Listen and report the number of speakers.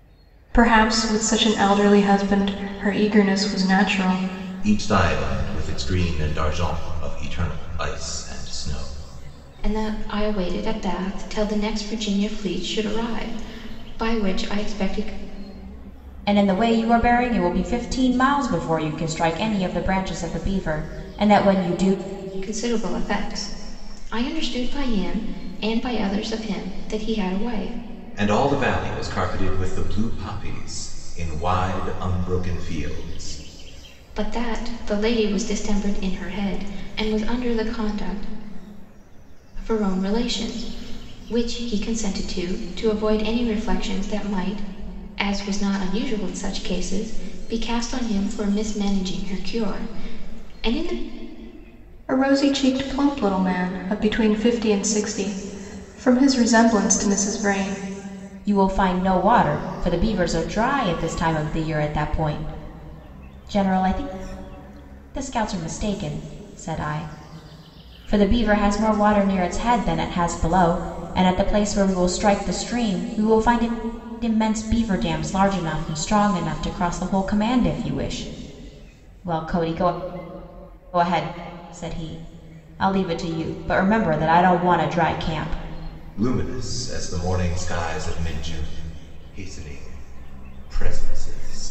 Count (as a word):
four